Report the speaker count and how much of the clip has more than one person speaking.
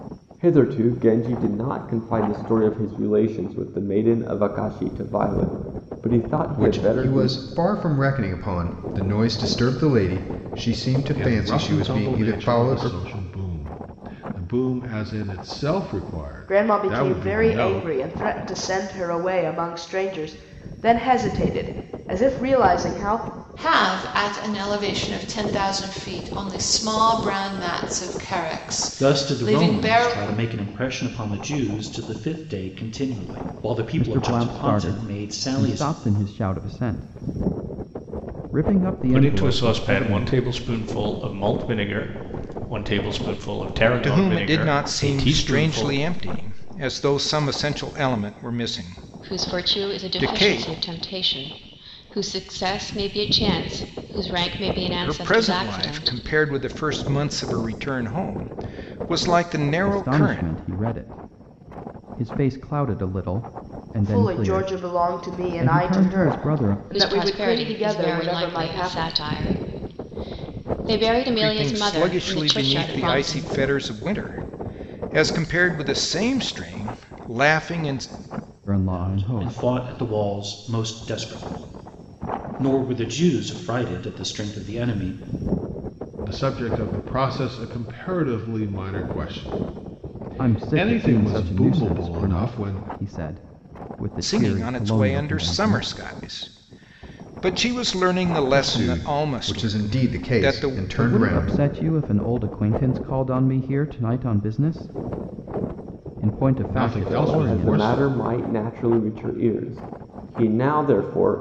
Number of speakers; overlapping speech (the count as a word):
ten, about 28%